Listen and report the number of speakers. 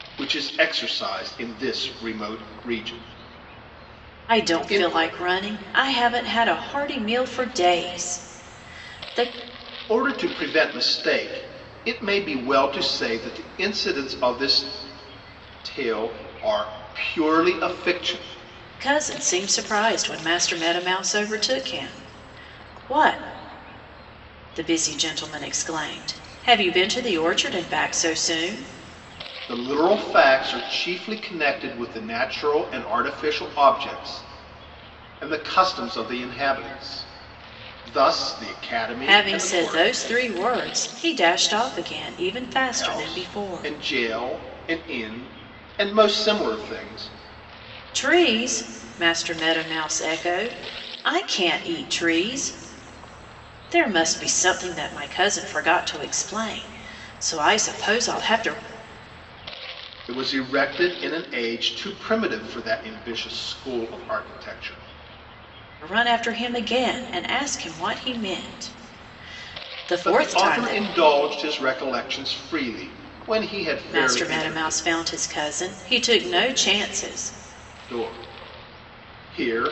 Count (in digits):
2